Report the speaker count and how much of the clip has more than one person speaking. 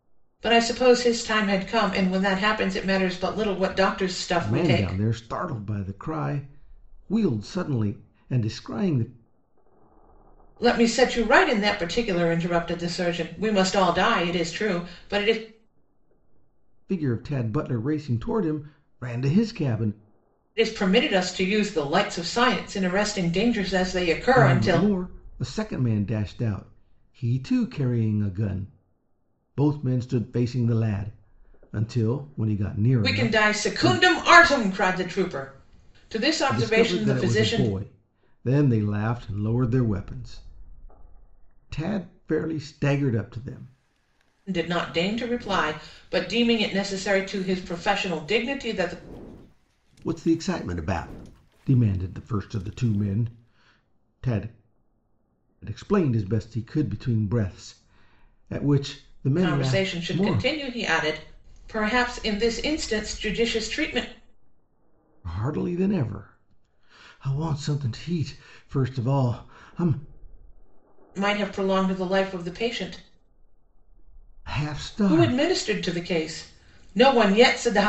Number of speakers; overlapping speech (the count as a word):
two, about 7%